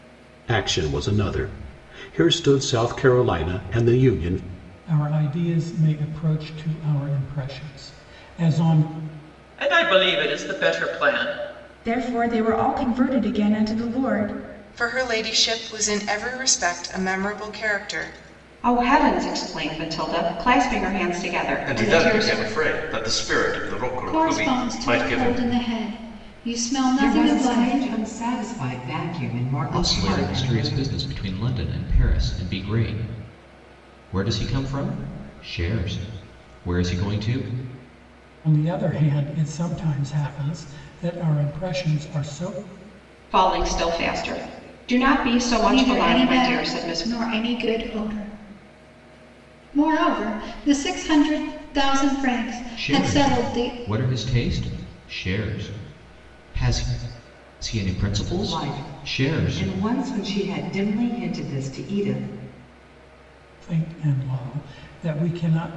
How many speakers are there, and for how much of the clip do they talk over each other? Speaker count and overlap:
ten, about 12%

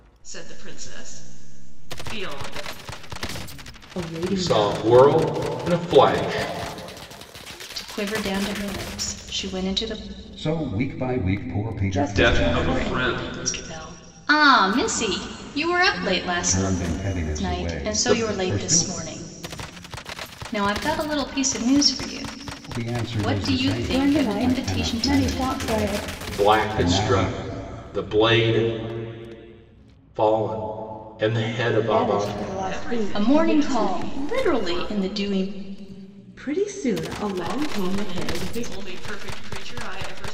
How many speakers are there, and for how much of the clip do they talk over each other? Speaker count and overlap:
seven, about 34%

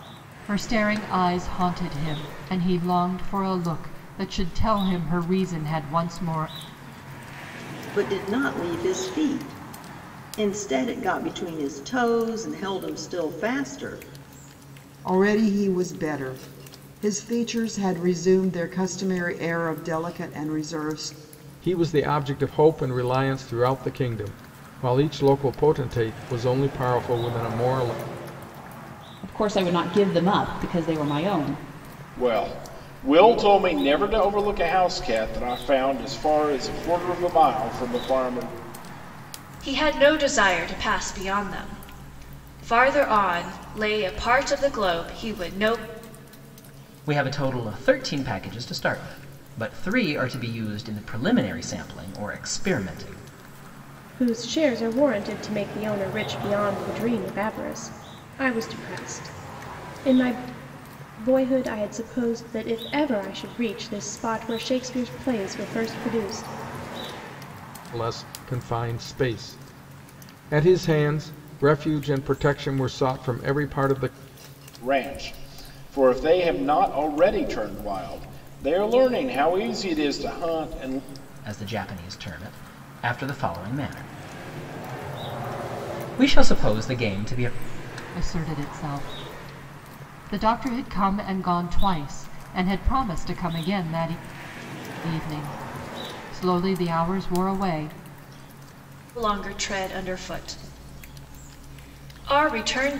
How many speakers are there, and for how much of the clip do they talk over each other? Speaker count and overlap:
nine, no overlap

